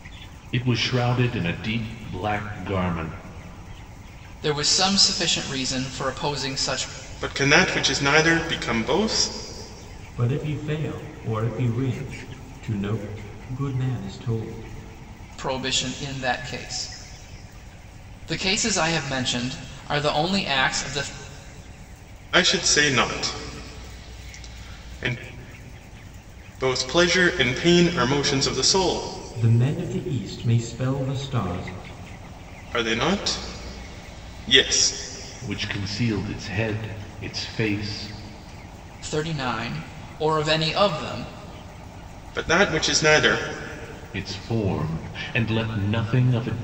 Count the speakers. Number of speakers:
4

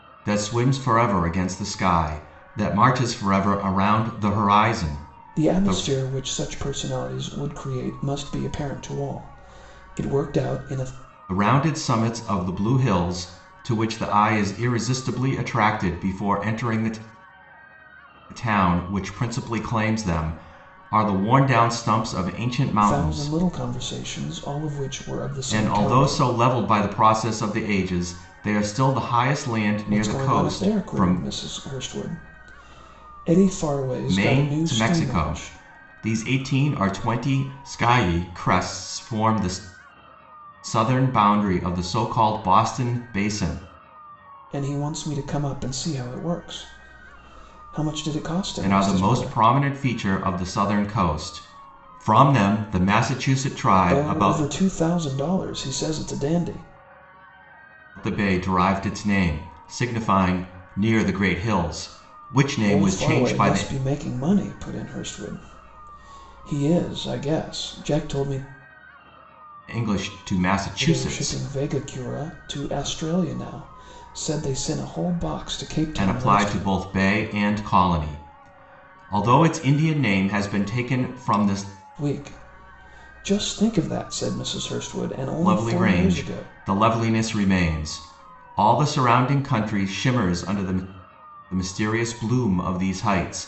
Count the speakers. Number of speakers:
2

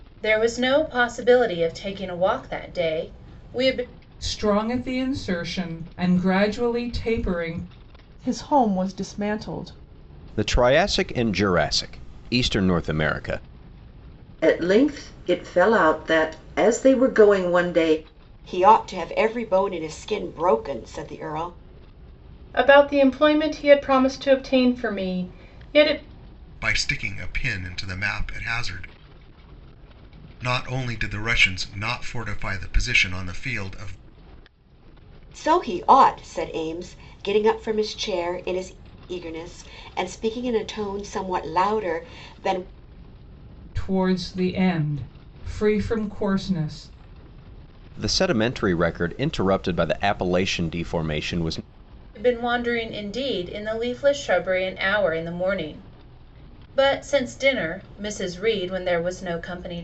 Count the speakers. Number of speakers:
8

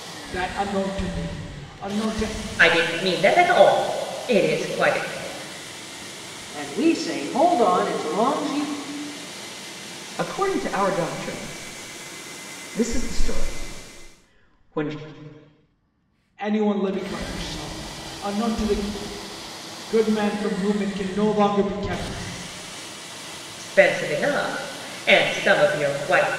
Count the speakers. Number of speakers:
4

